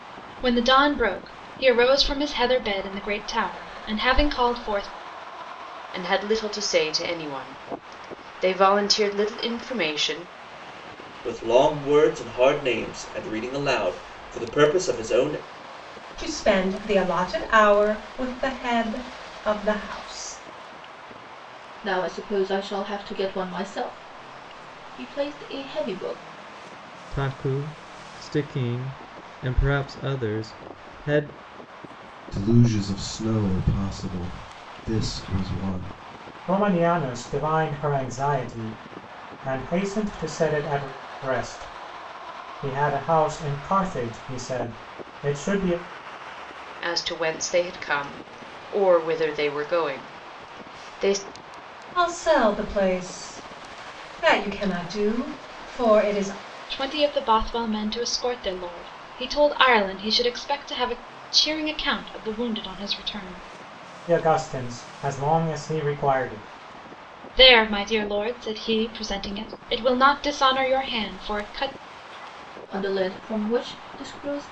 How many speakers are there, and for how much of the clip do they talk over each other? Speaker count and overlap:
eight, no overlap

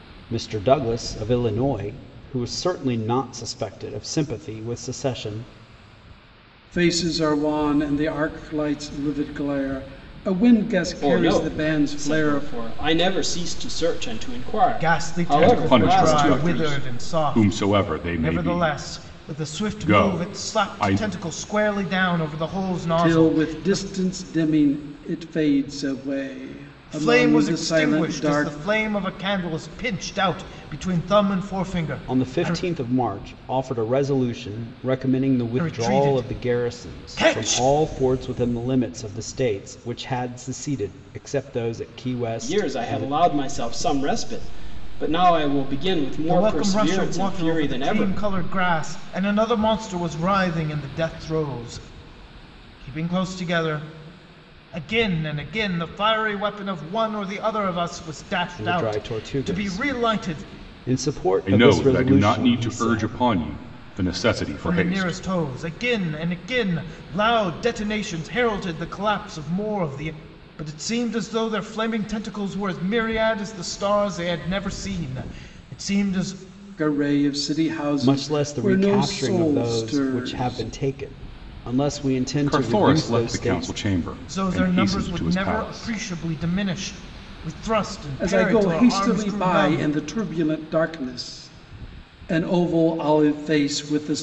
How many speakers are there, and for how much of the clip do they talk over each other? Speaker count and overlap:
five, about 29%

